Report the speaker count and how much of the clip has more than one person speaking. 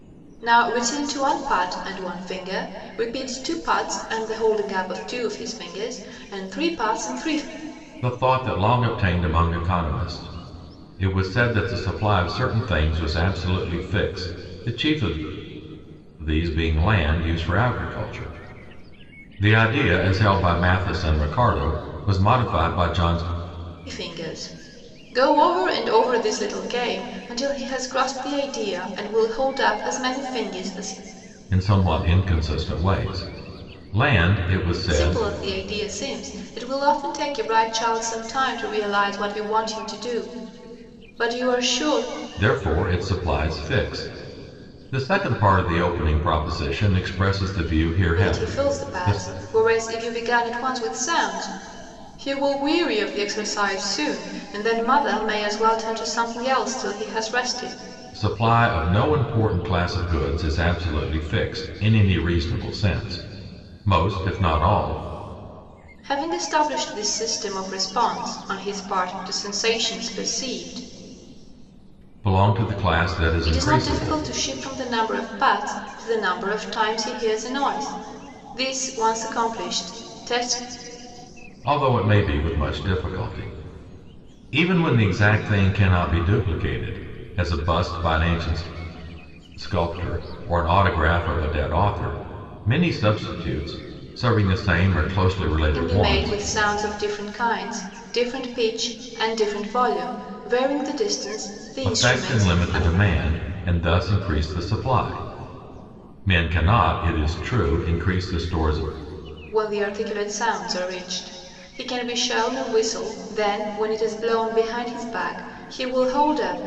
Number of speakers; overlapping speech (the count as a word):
two, about 4%